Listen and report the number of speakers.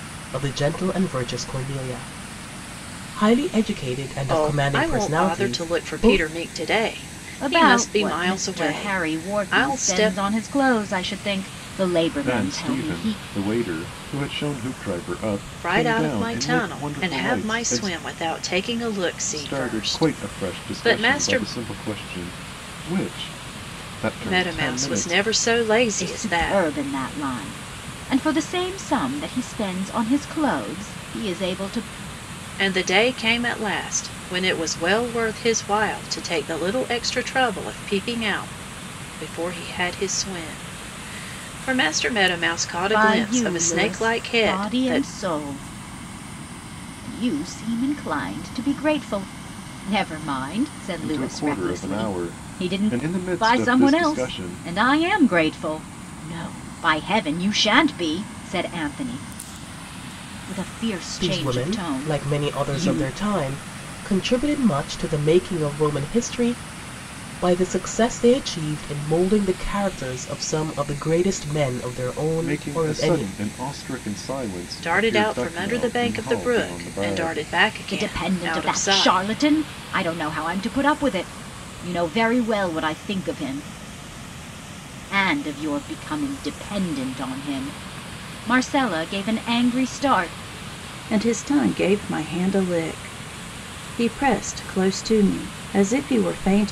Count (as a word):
four